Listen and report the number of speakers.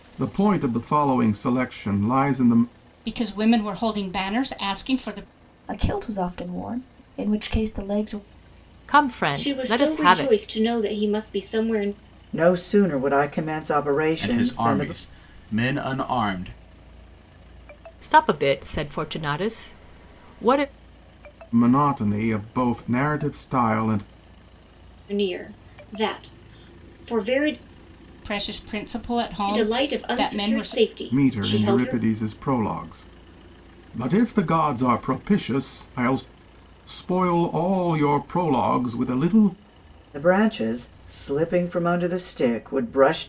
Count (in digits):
7